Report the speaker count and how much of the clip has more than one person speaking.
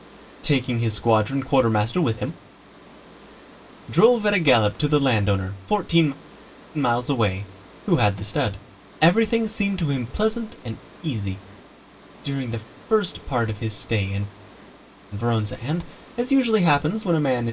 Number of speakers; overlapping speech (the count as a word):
one, no overlap